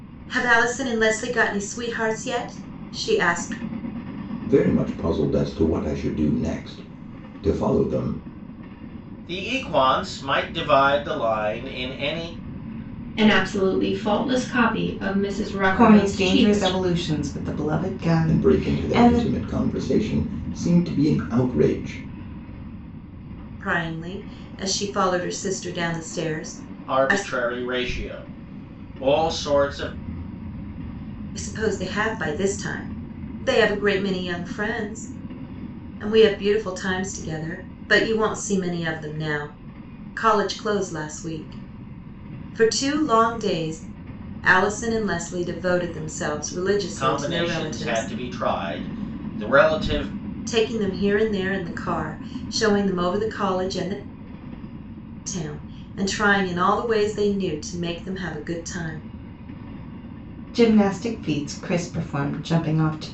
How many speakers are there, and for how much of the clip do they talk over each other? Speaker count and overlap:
five, about 6%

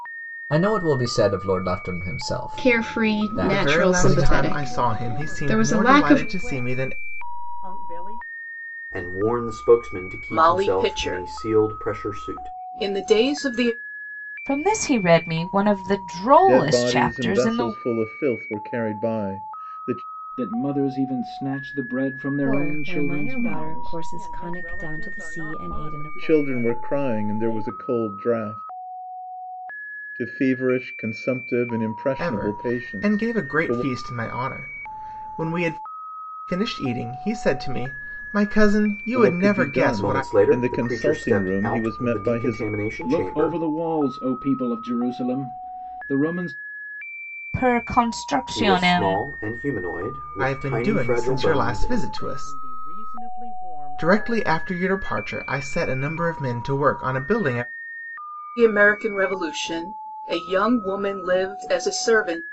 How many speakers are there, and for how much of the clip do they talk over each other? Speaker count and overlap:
ten, about 36%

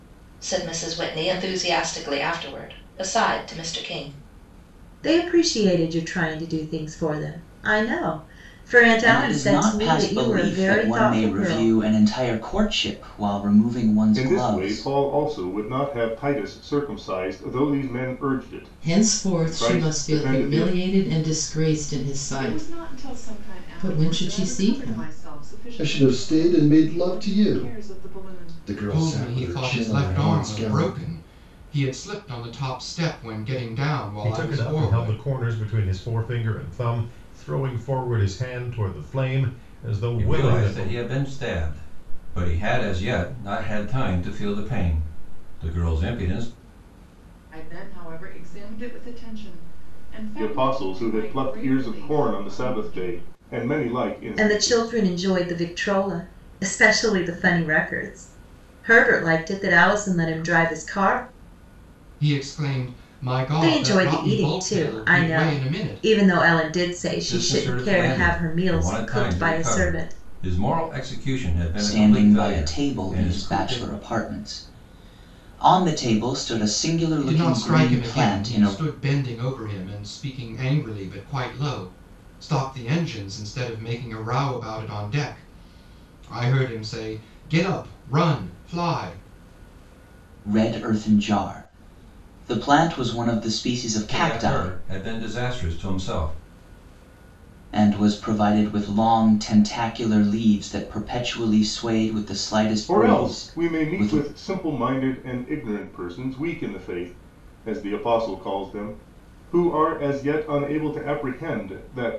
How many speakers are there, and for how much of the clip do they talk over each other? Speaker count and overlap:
ten, about 27%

